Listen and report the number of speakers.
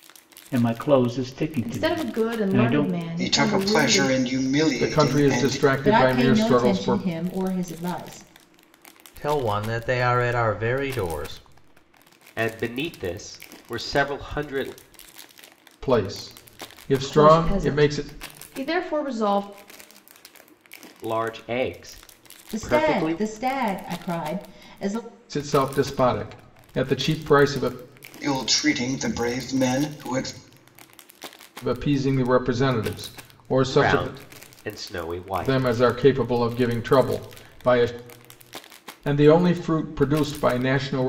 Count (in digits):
7